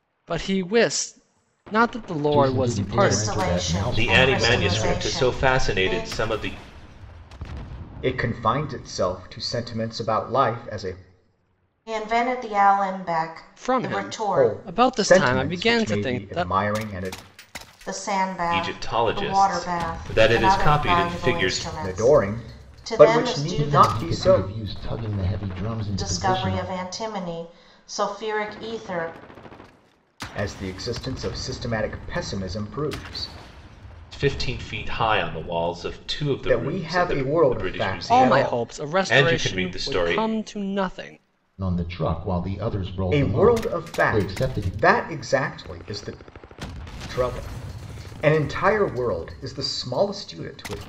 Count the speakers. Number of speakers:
5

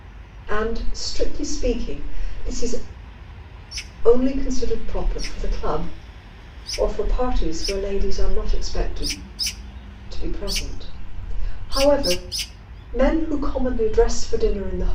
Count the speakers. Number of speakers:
1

